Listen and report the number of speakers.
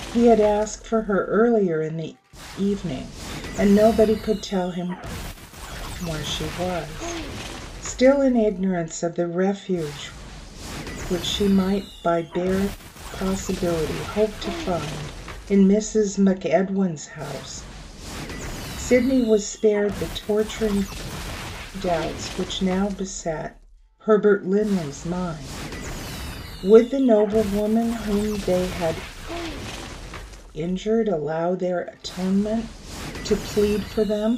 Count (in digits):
1